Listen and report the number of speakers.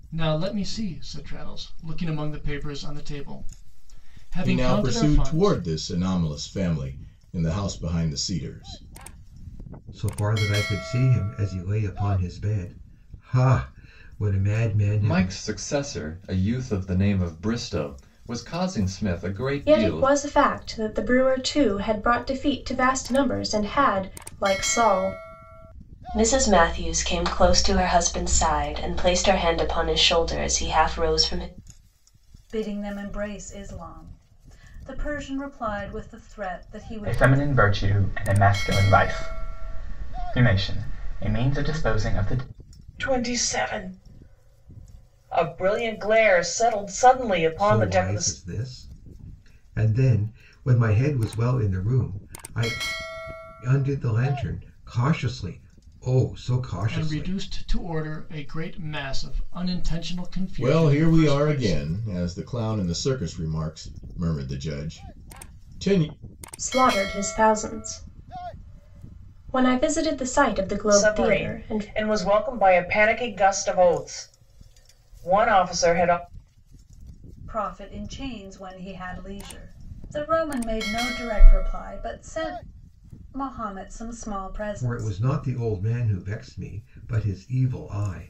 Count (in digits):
9